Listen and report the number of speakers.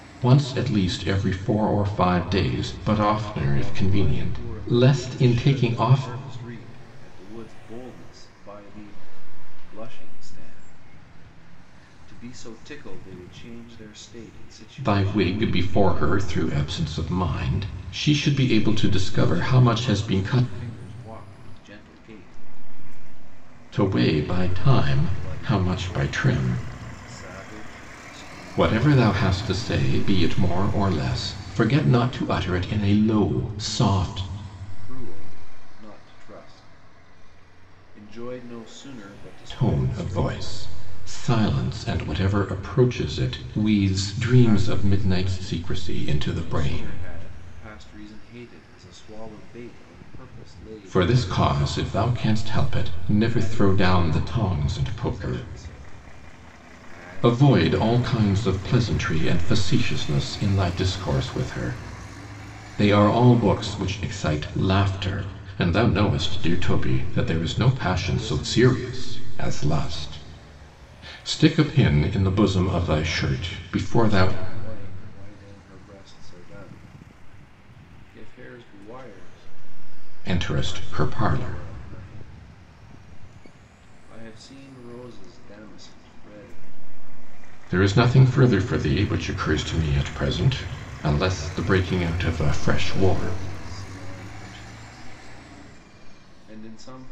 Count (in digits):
2